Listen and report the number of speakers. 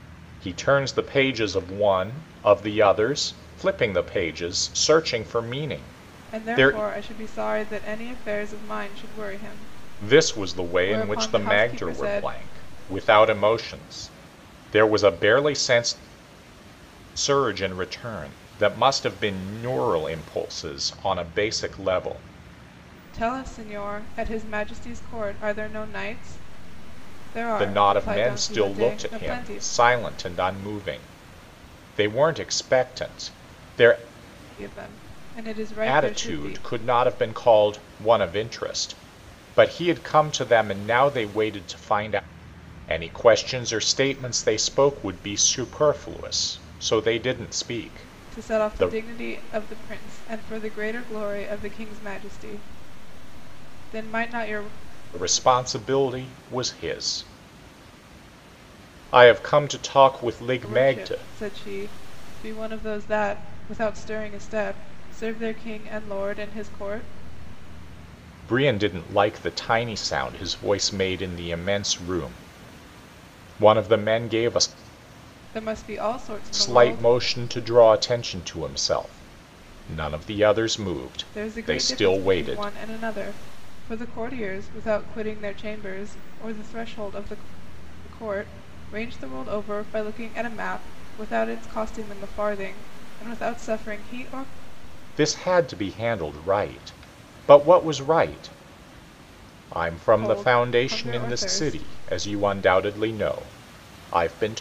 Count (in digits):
2